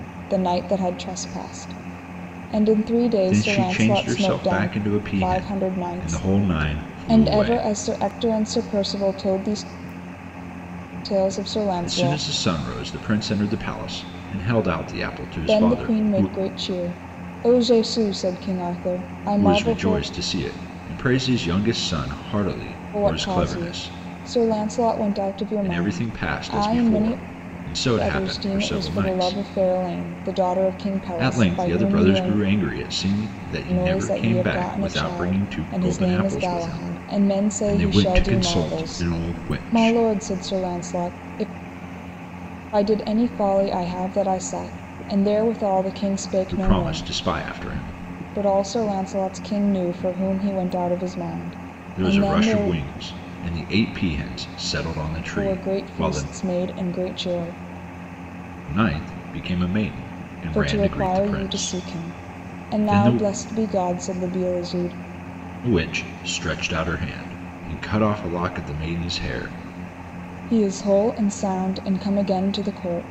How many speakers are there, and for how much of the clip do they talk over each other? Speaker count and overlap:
2, about 31%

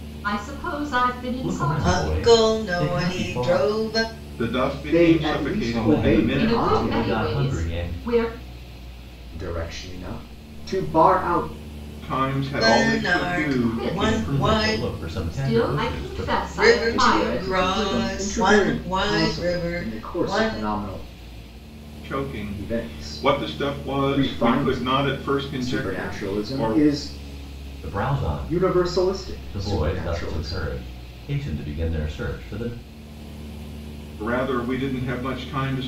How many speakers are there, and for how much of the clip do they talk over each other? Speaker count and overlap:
5, about 52%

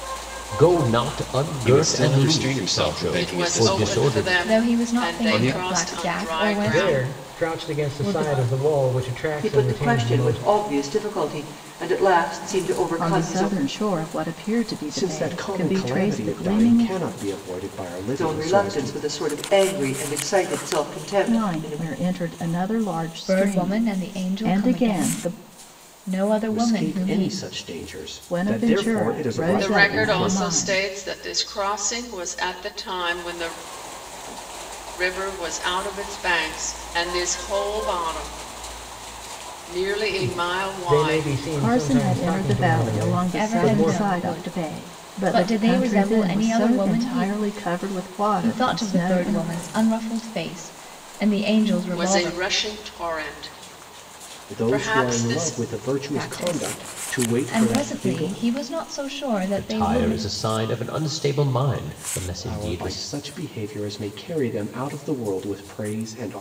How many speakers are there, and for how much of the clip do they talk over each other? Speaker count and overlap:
8, about 47%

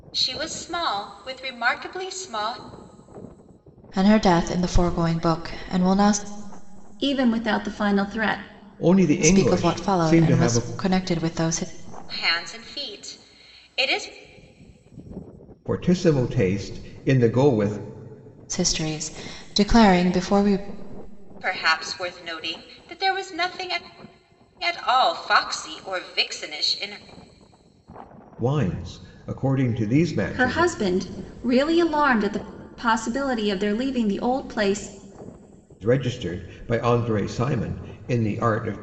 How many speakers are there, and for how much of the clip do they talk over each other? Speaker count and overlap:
4, about 5%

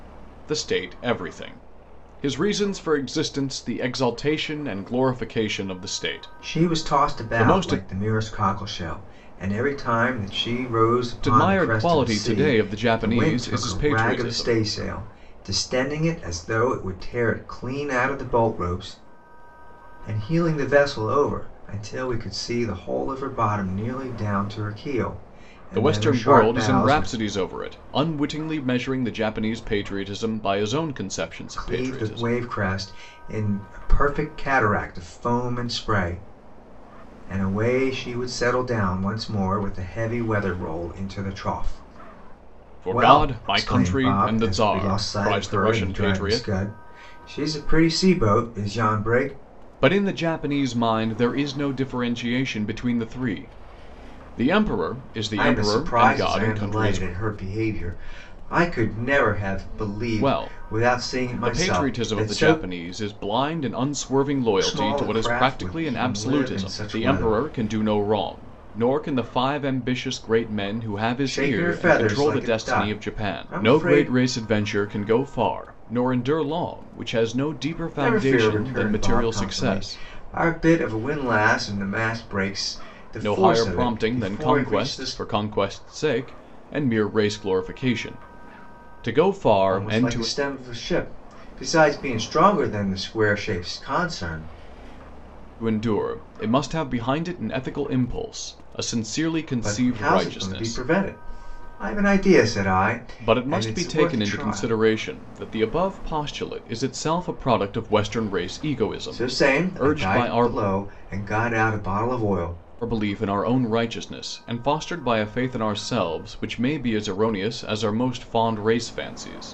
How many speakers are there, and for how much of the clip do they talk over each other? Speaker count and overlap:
2, about 25%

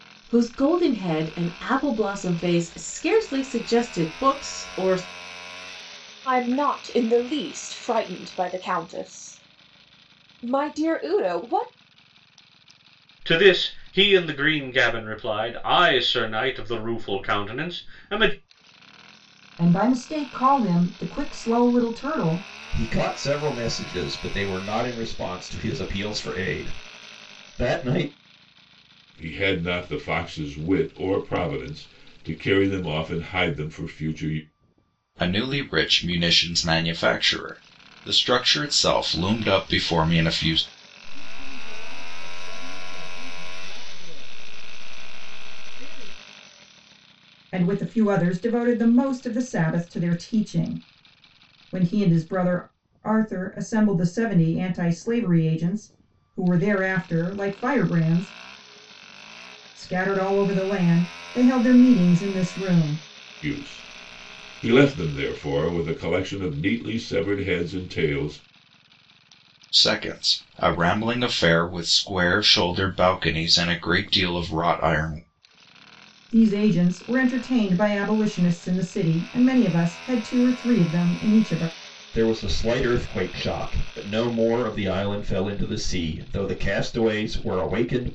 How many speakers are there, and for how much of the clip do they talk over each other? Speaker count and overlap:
8, no overlap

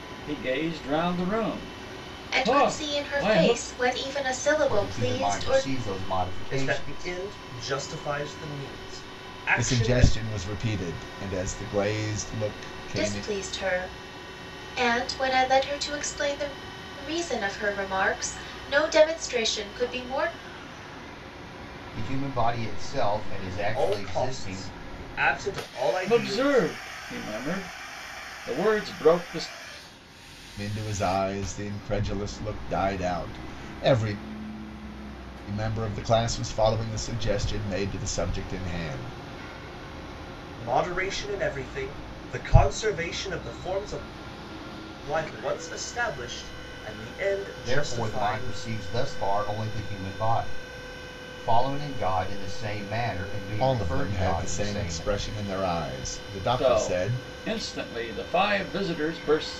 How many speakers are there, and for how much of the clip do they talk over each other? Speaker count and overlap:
5, about 15%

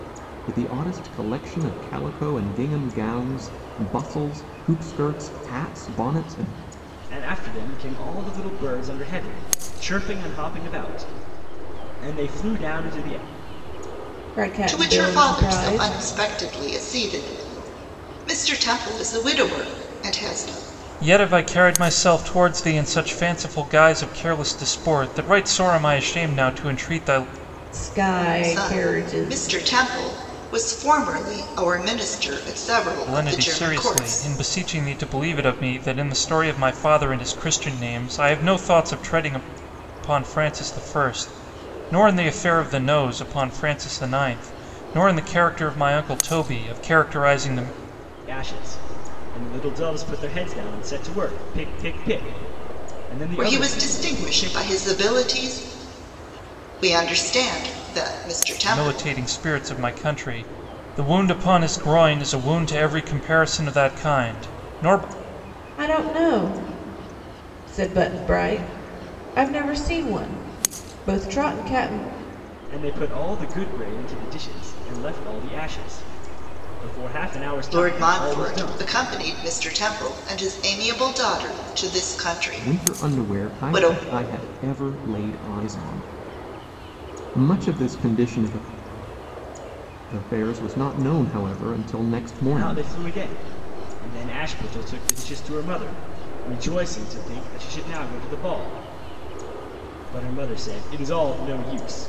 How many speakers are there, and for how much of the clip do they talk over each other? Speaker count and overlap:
5, about 8%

